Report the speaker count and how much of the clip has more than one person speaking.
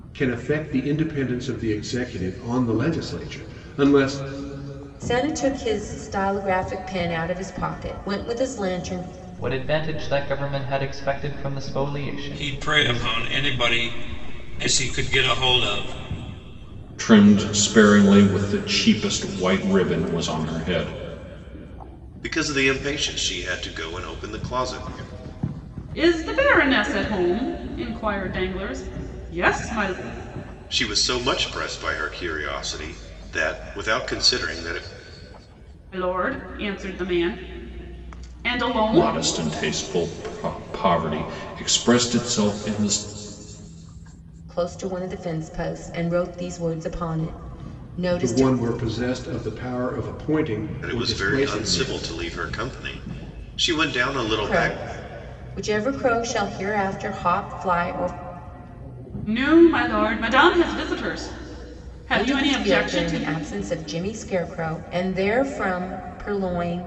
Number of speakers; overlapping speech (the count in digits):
7, about 7%